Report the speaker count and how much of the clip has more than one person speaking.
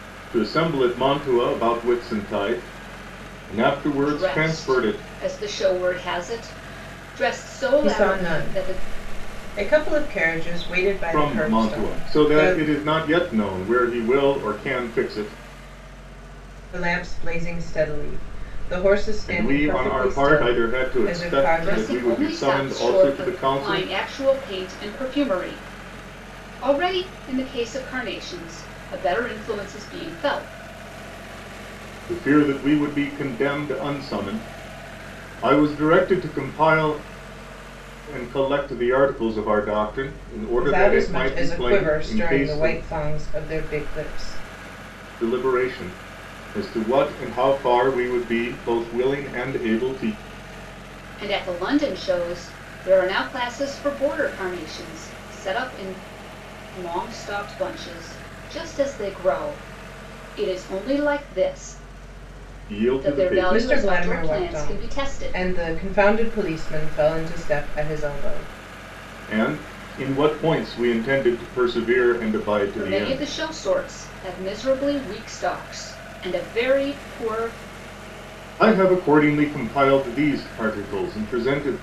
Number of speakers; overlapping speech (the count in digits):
3, about 17%